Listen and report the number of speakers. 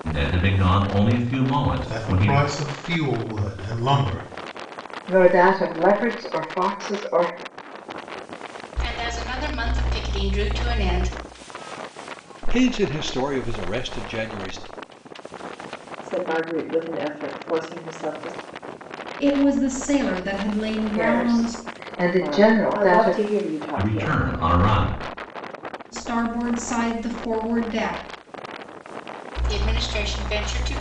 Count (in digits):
7